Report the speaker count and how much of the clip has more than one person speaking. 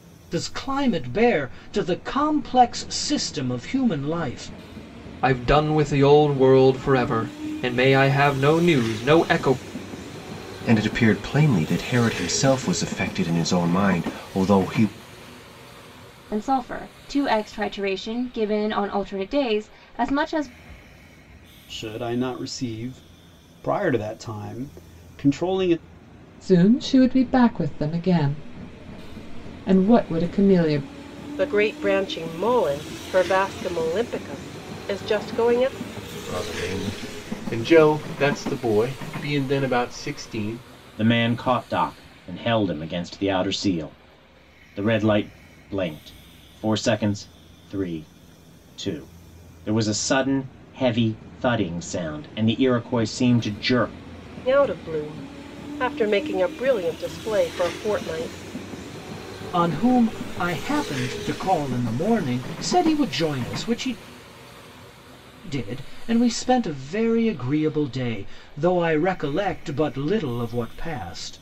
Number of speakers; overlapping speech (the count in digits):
9, no overlap